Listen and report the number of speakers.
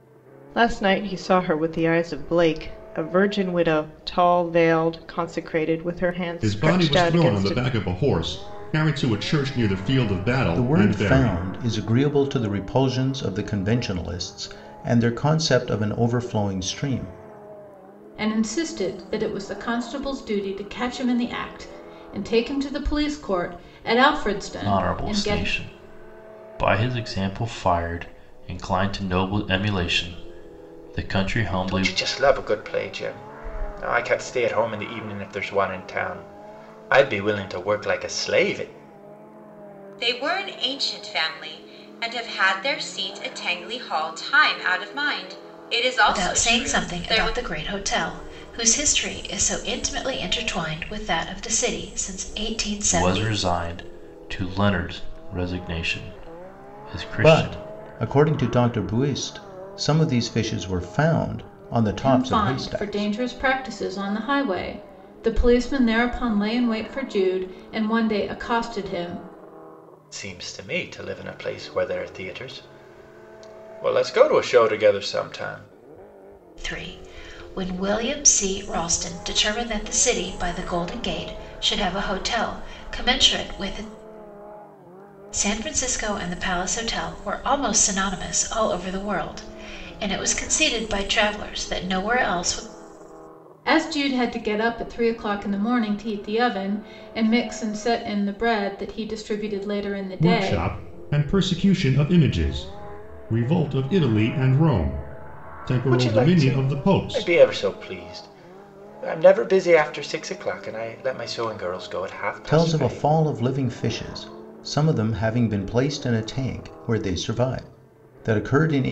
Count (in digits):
8